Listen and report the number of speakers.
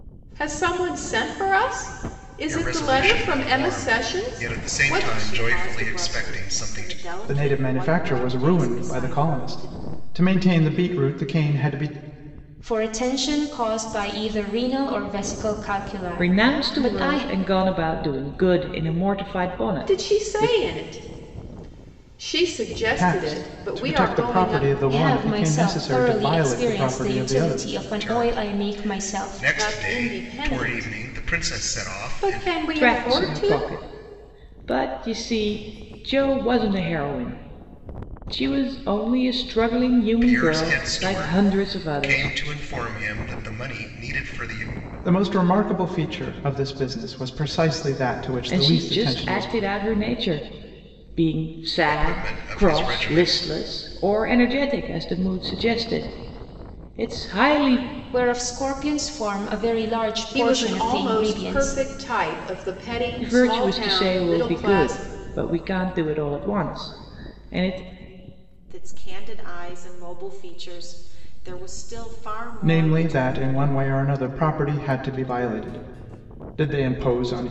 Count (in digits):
6